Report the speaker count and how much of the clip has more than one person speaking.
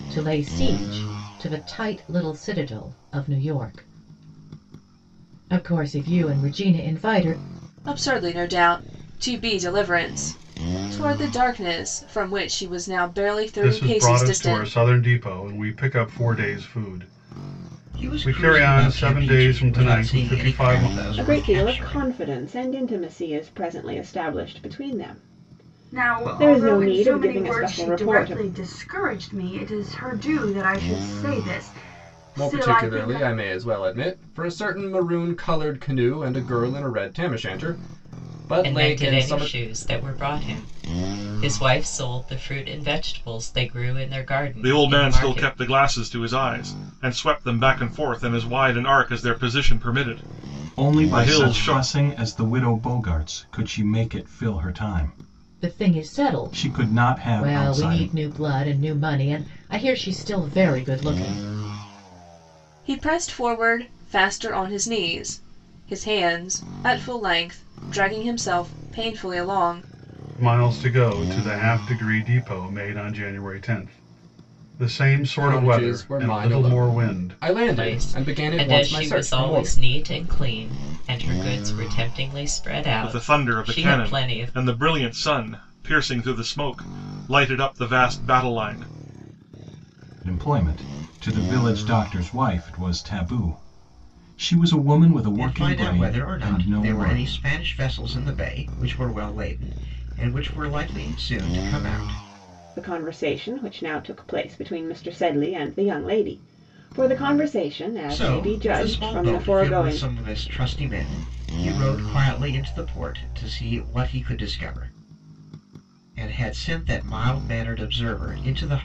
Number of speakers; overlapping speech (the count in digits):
10, about 21%